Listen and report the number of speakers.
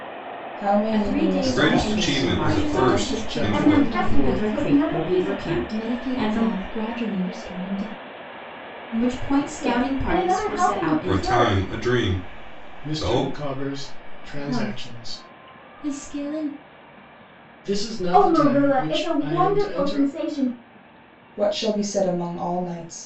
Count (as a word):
six